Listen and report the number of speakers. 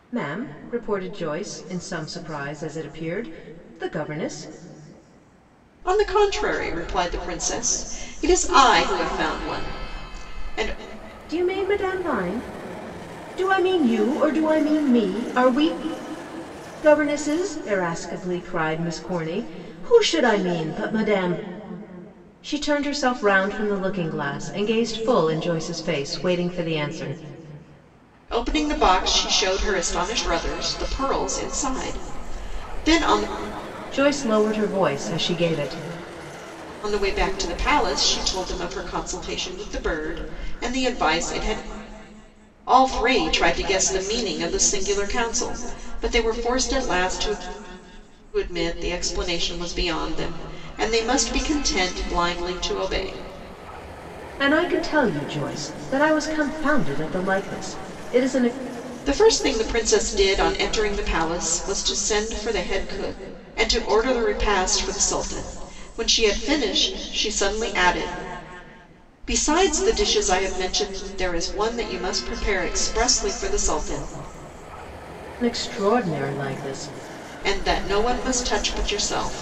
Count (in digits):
2